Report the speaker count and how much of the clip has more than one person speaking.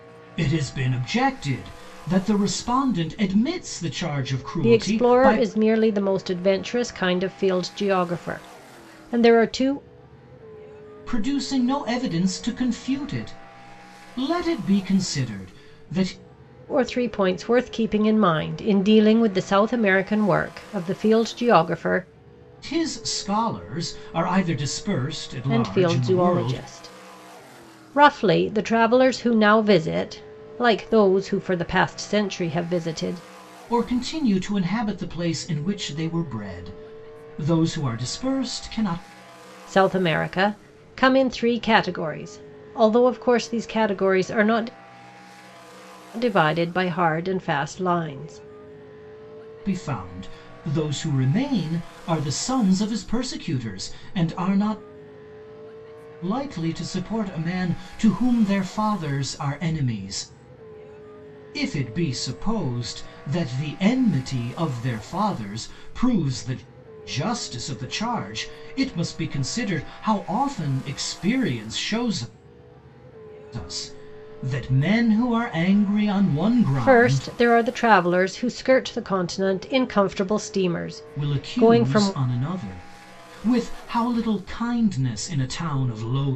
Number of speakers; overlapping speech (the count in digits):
2, about 4%